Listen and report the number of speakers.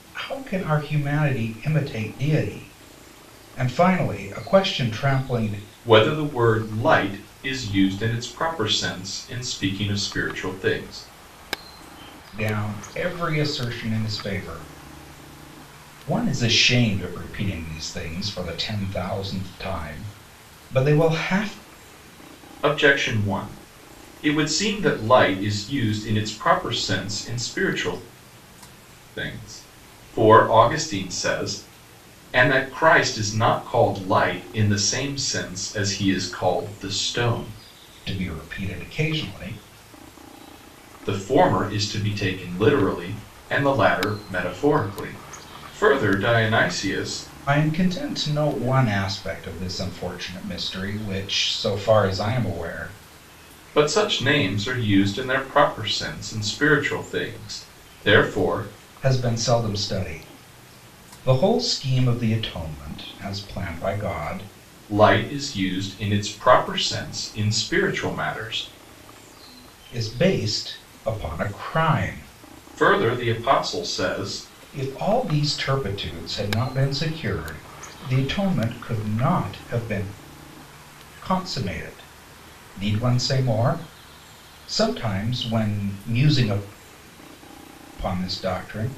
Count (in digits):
2